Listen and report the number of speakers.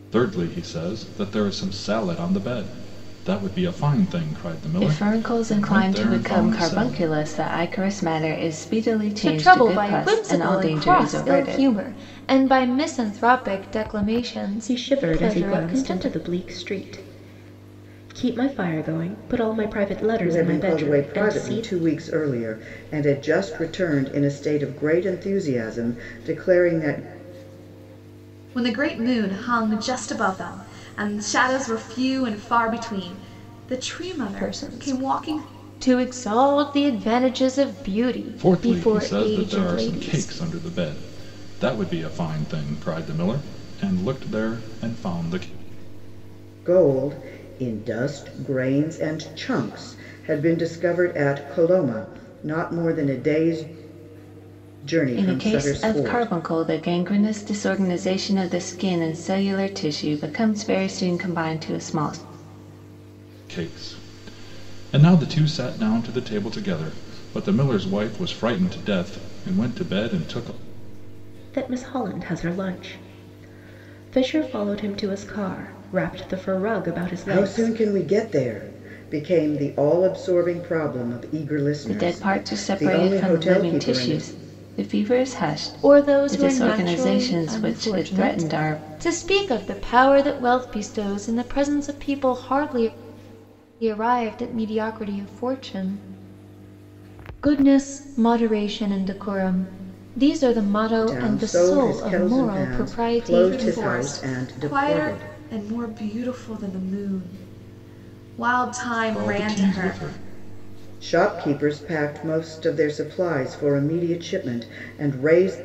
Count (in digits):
6